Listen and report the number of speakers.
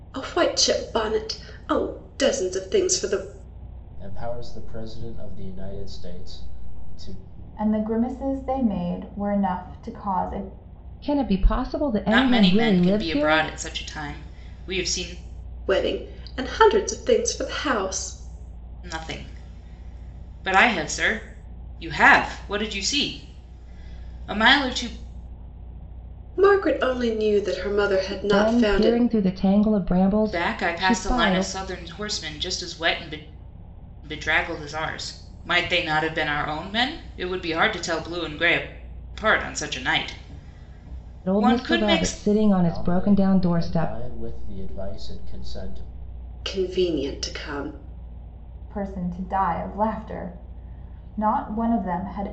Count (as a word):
five